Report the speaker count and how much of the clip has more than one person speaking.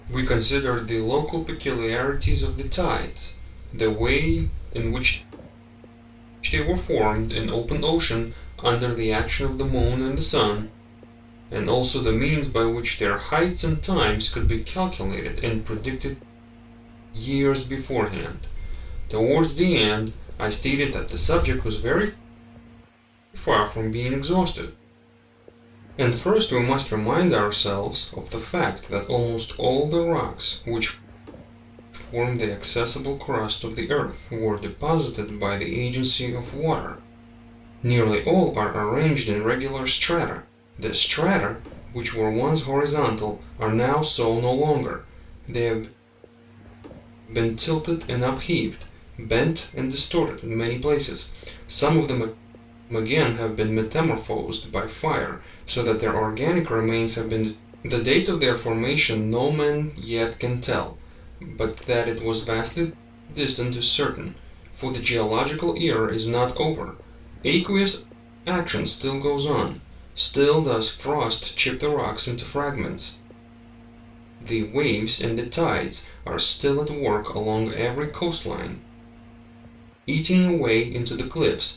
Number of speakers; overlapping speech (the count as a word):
one, no overlap